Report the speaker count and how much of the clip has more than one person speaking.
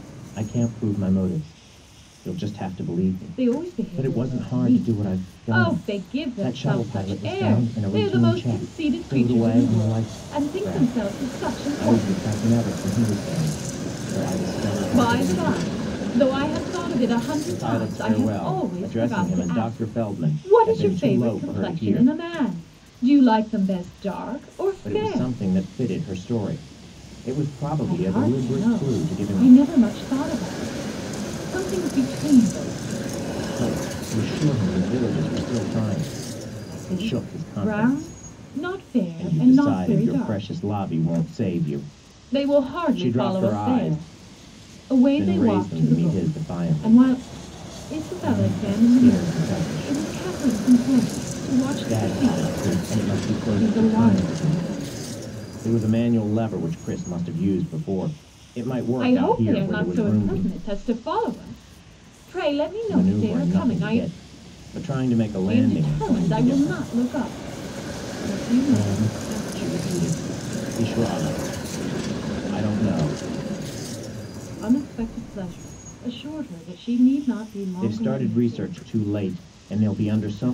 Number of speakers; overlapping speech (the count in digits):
2, about 41%